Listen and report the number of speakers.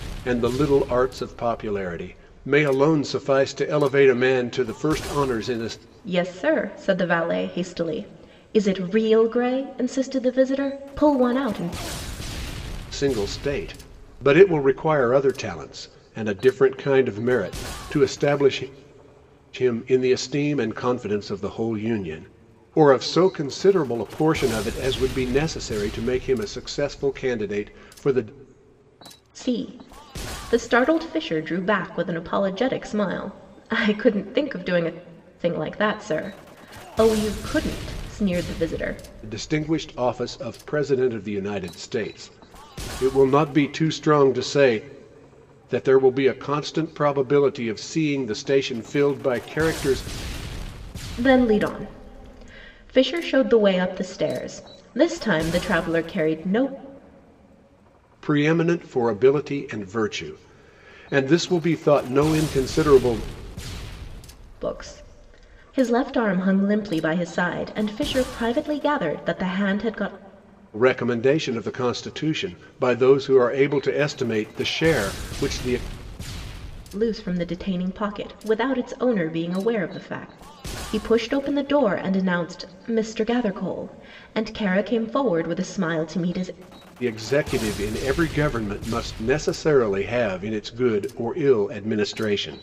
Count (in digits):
2